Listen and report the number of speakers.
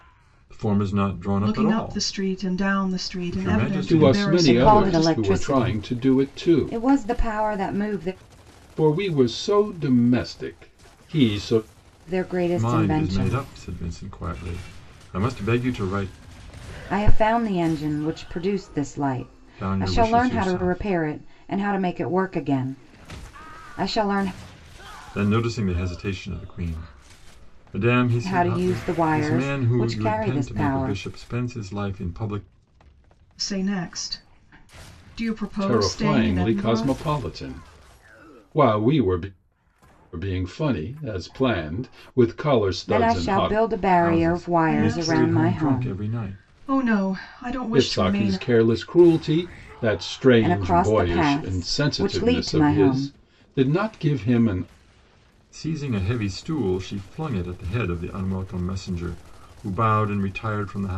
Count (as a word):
four